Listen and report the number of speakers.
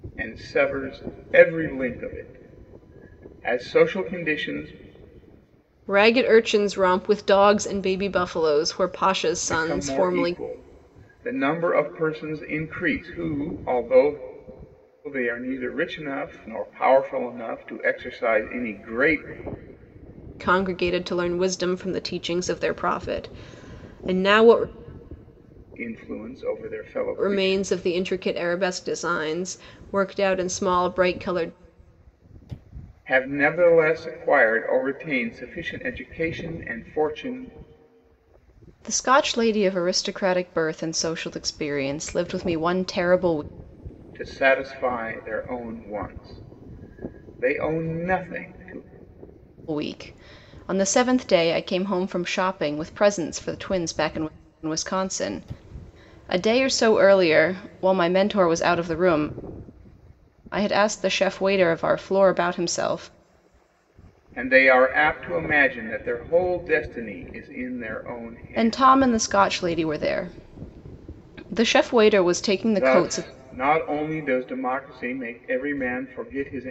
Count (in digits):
2